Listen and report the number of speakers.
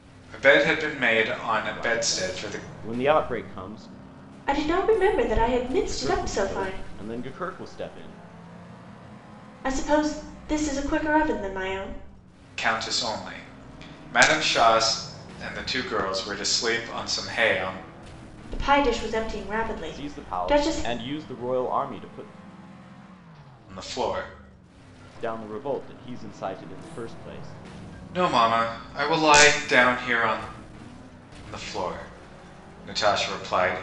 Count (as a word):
three